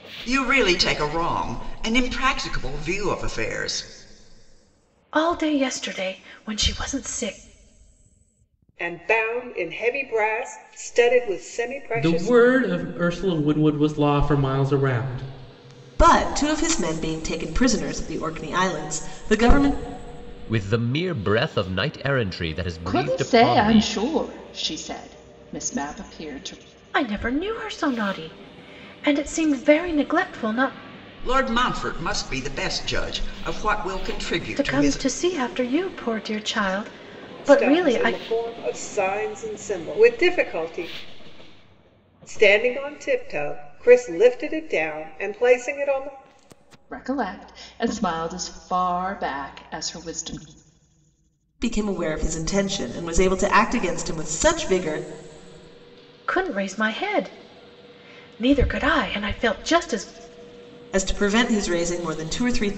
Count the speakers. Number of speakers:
7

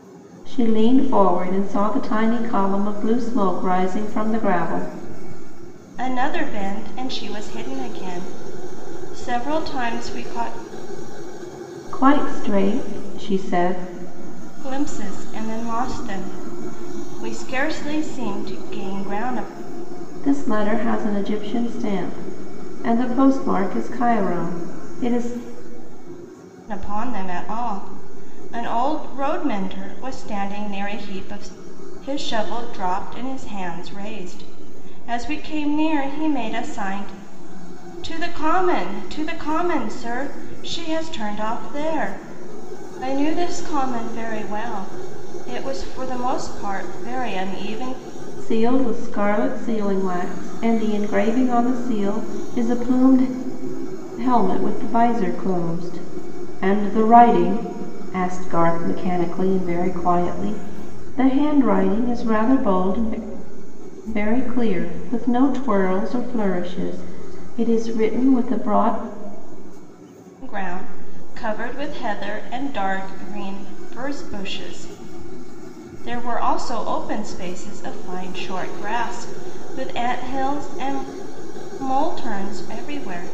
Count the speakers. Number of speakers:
2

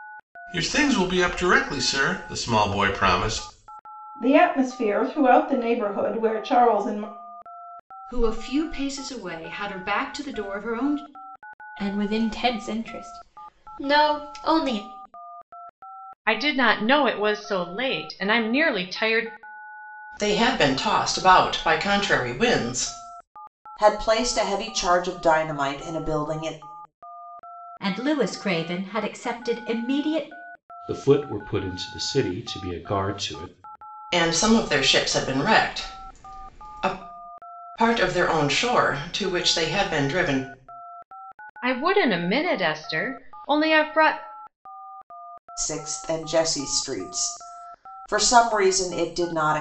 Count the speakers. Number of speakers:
9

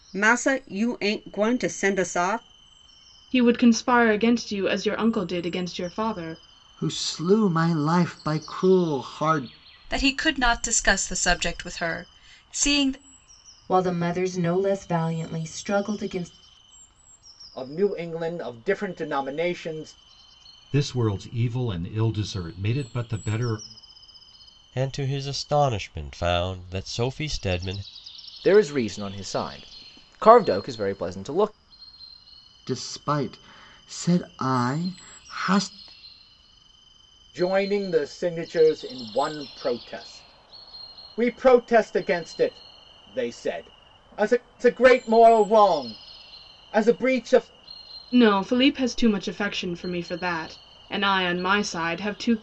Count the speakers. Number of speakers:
9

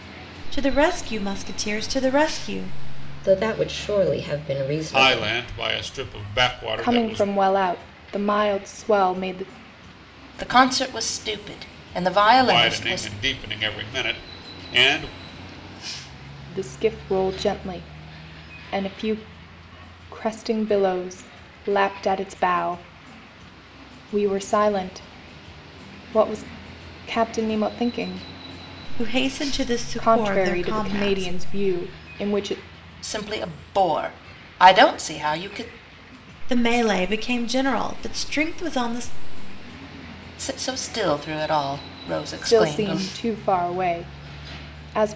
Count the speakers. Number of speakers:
5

